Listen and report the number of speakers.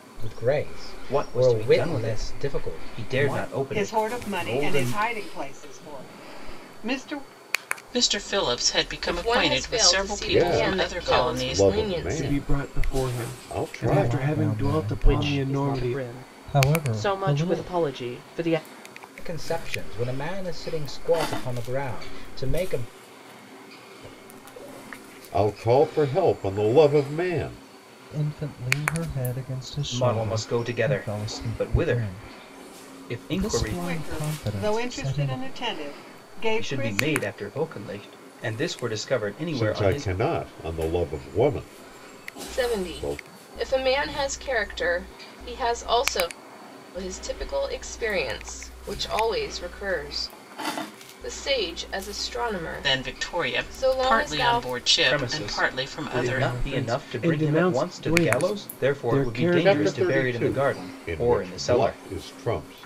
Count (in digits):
9